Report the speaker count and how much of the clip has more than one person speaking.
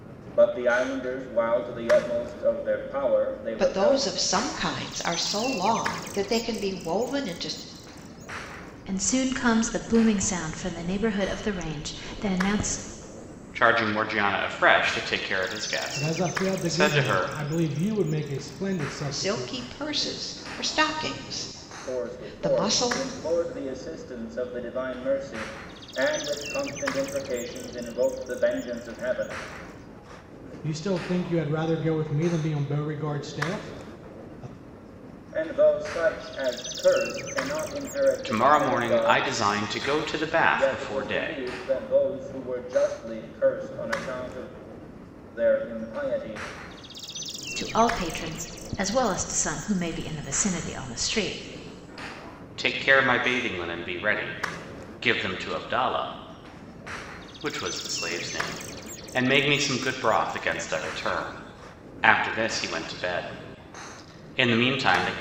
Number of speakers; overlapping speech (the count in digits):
5, about 9%